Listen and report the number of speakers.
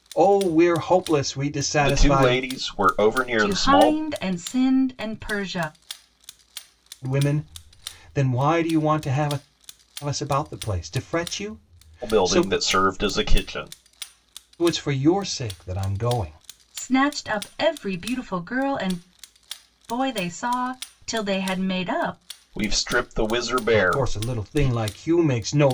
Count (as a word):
three